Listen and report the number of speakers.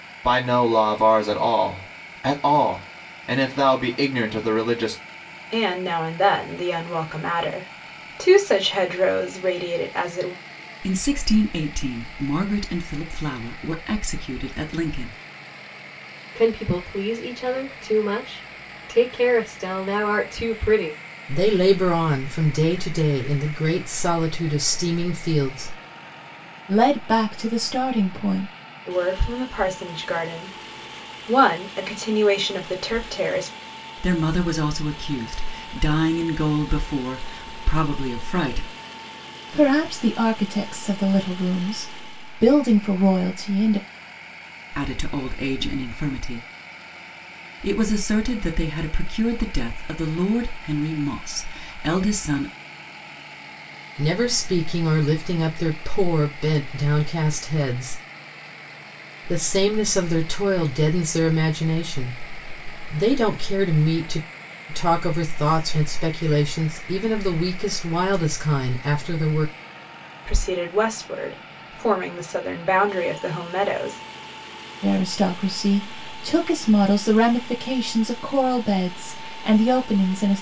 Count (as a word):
six